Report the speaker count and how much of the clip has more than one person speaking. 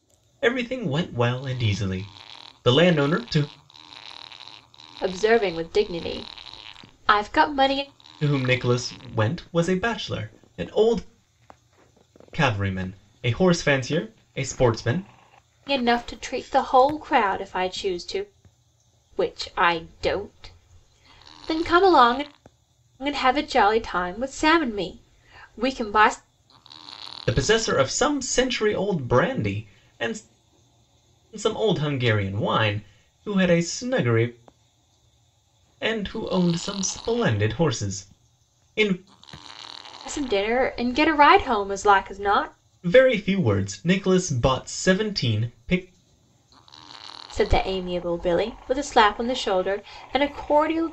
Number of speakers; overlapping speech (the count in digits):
2, no overlap